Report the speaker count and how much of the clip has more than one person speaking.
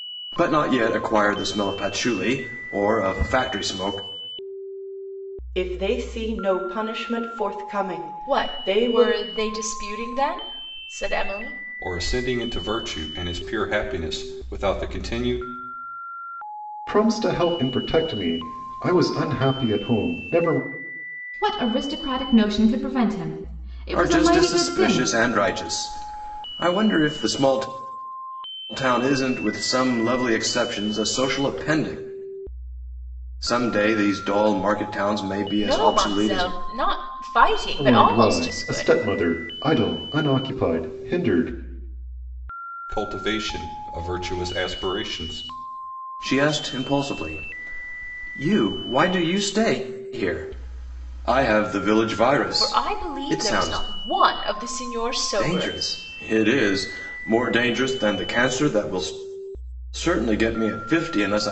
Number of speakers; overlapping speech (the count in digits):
6, about 10%